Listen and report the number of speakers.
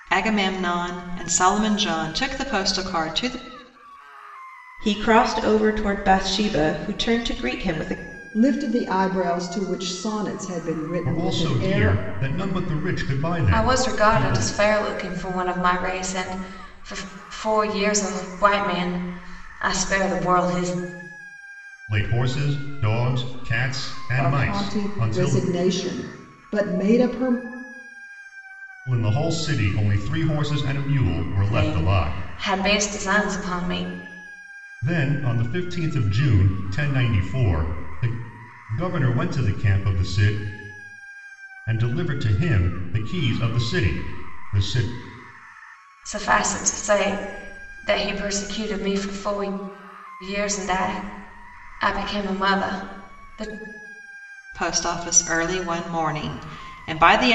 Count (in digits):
5